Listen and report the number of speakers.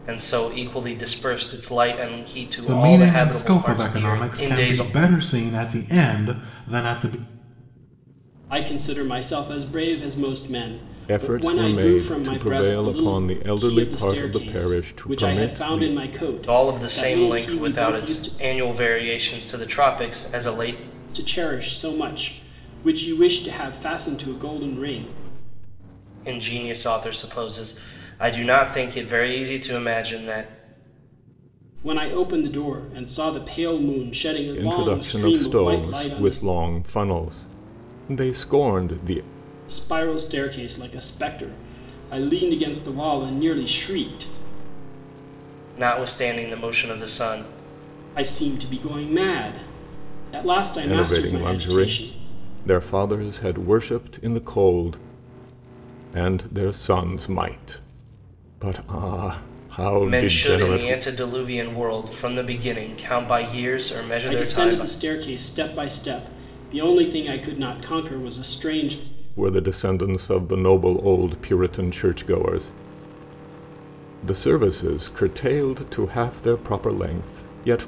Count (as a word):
four